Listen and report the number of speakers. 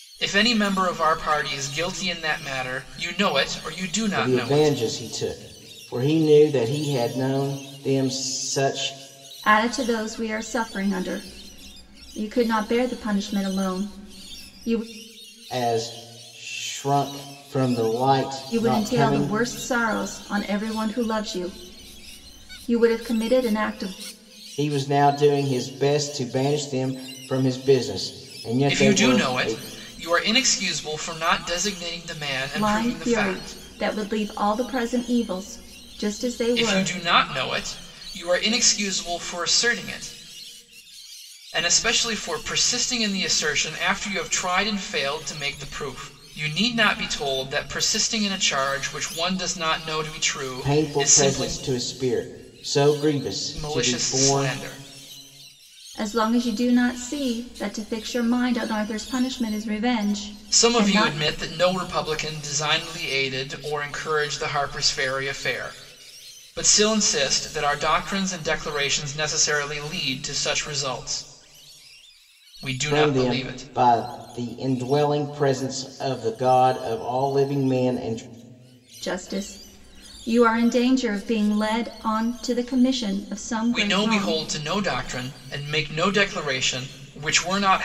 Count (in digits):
3